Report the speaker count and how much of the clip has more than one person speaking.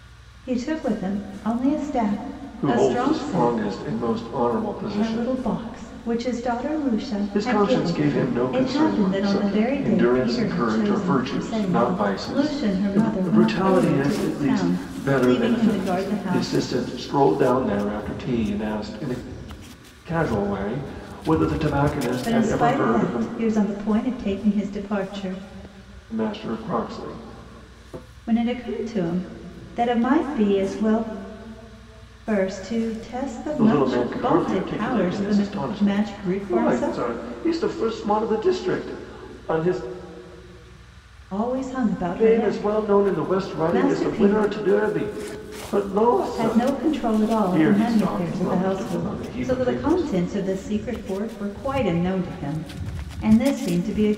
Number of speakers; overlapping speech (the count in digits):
2, about 40%